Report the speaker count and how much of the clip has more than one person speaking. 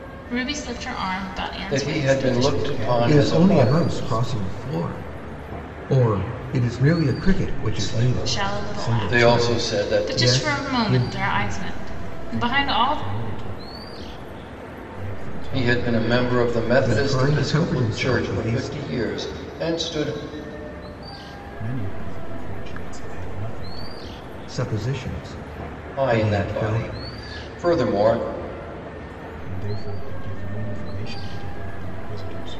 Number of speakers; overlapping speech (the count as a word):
four, about 40%